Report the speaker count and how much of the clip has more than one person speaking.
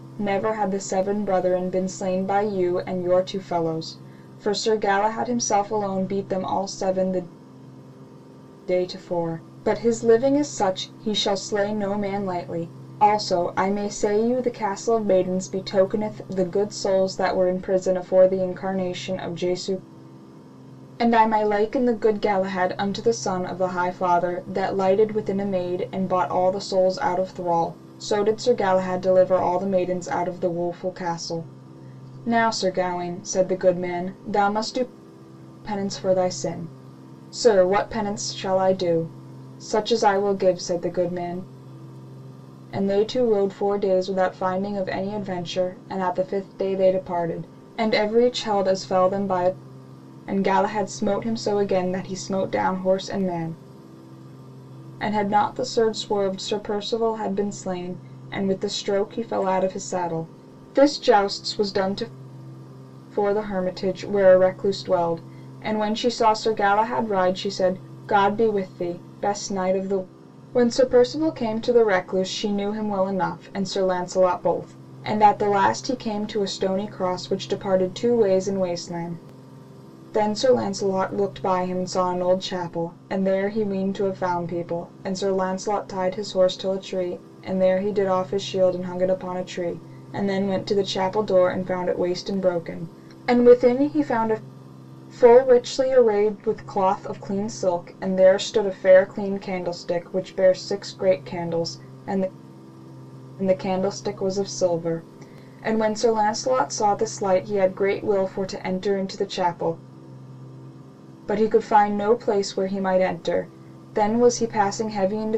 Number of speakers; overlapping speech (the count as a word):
one, no overlap